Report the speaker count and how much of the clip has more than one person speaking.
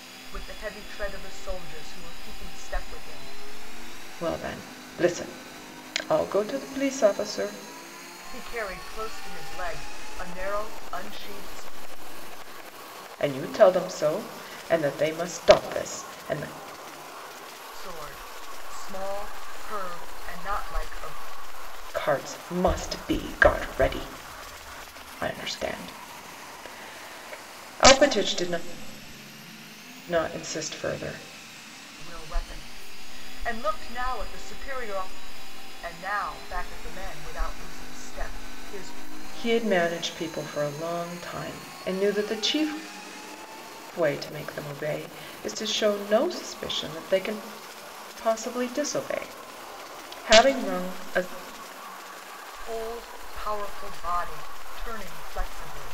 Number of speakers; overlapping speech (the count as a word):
two, no overlap